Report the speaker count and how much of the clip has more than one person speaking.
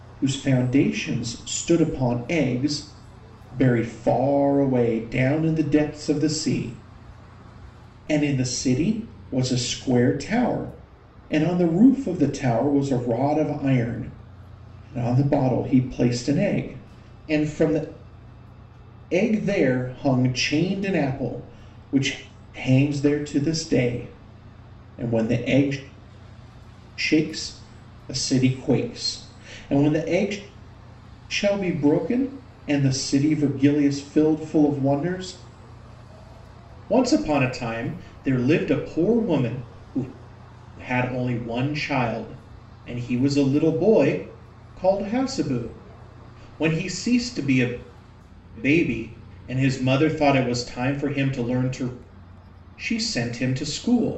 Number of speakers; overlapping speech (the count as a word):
one, no overlap